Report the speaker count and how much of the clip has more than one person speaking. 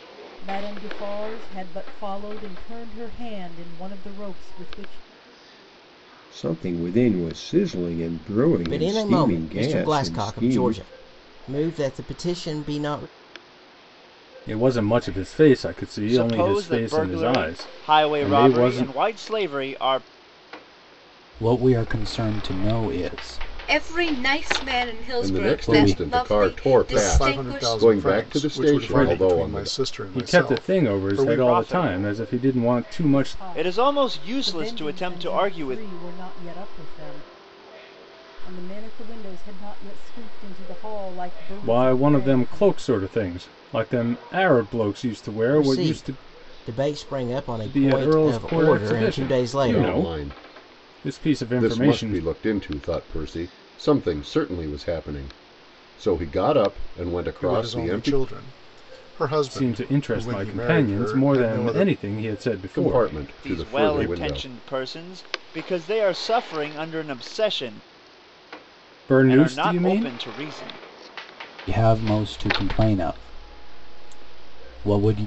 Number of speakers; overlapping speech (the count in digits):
9, about 39%